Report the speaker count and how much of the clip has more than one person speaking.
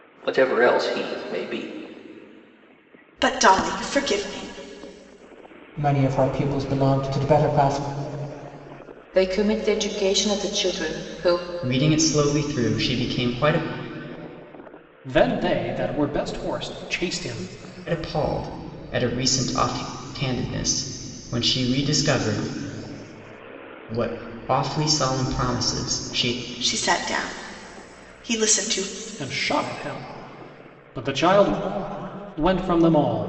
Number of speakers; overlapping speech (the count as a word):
six, no overlap